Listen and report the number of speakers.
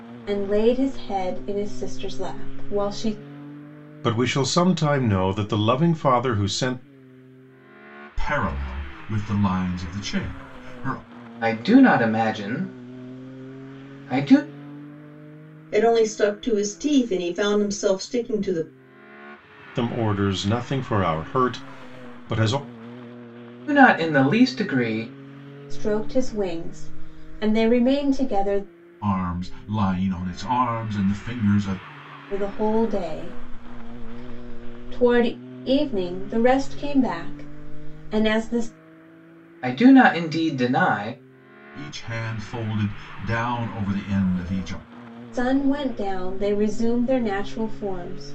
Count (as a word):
five